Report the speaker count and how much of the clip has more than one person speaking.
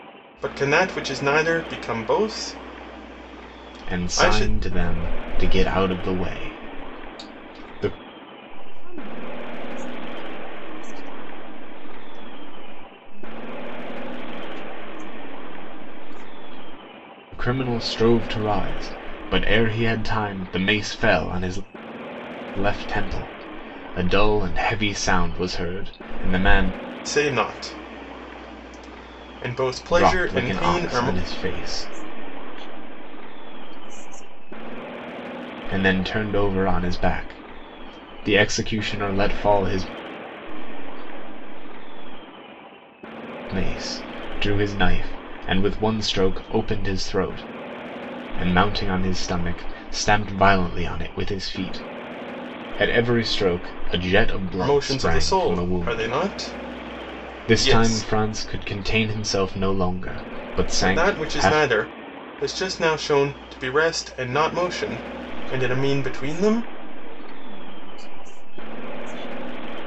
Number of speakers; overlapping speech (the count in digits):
3, about 10%